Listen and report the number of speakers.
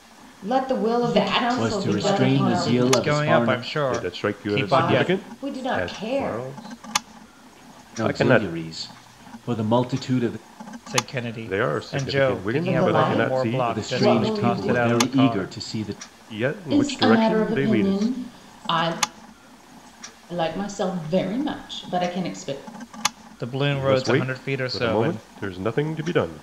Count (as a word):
five